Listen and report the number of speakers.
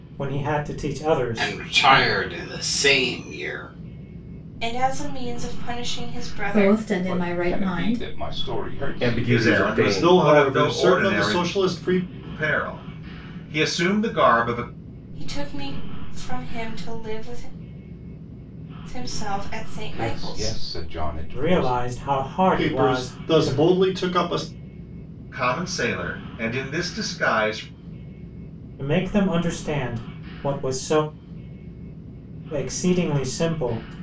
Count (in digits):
8